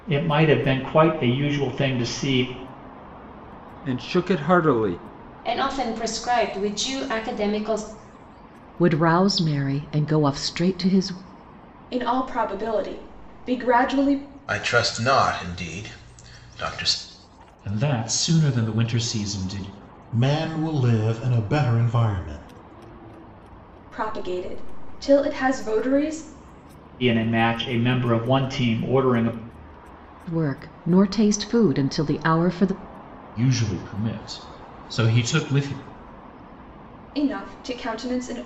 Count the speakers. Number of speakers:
8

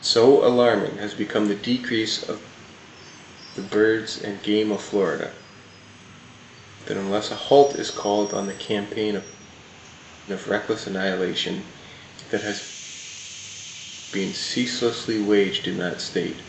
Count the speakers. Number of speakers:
1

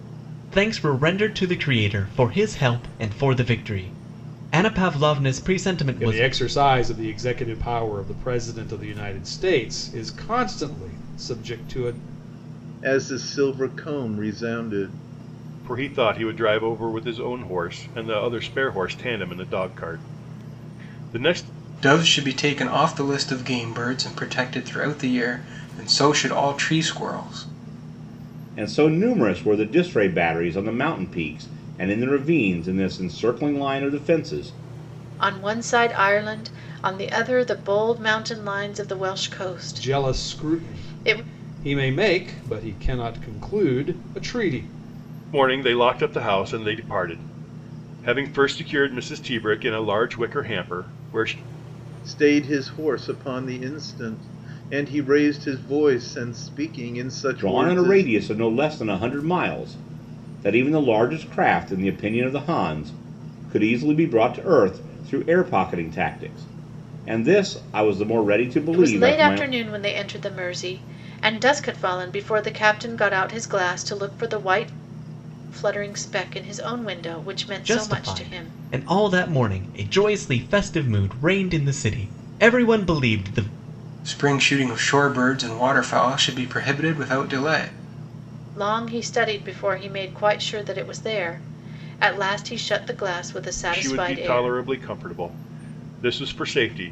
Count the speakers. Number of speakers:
7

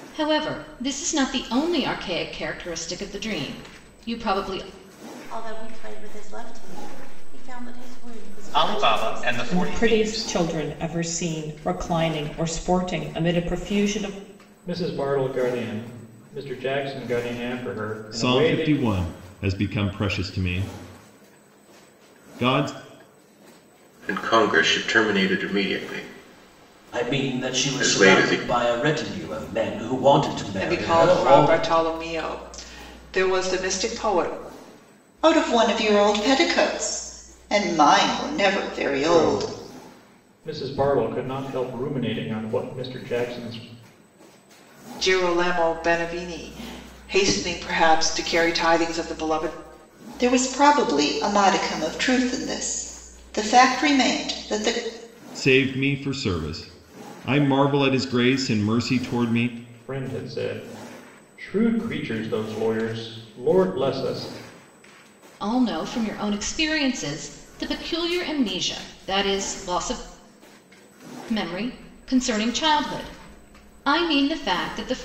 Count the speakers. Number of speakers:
10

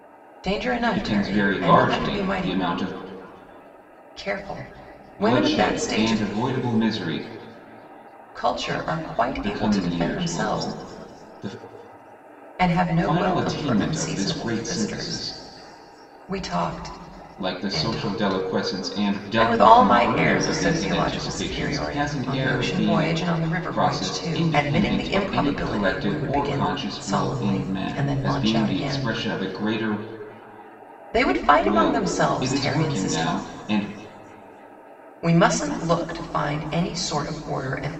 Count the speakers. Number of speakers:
2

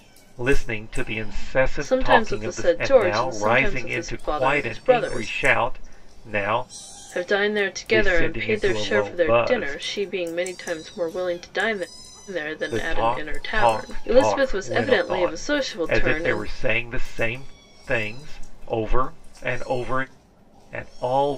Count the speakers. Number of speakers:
2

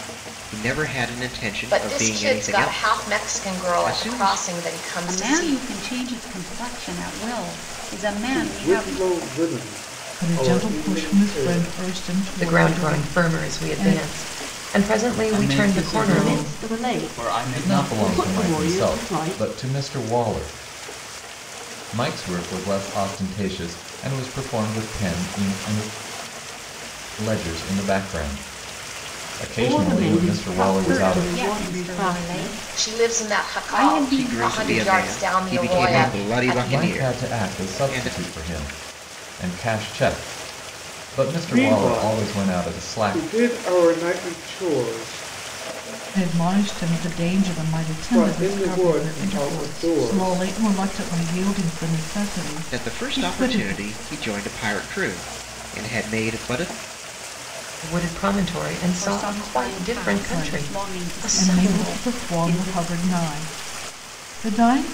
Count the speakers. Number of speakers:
9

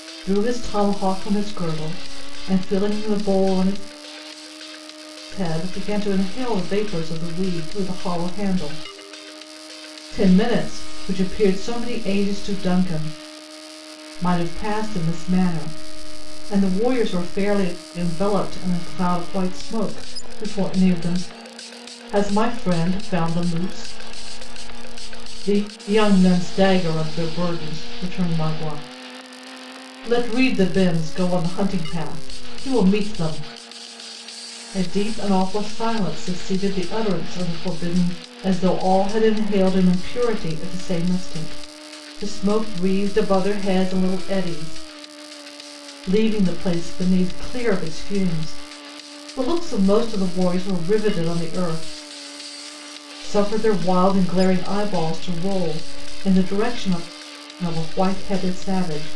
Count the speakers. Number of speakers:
1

